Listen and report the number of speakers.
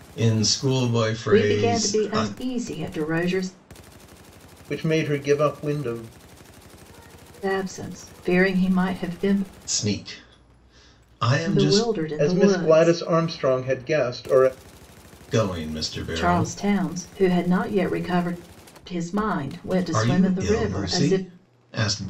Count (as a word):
three